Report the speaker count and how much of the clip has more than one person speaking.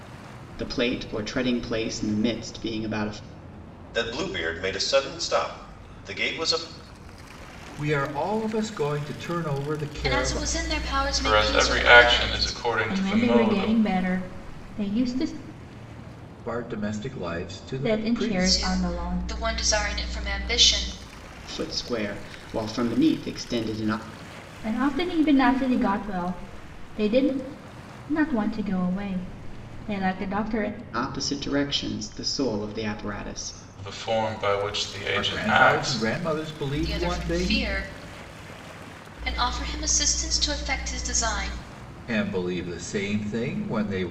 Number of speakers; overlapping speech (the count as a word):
six, about 14%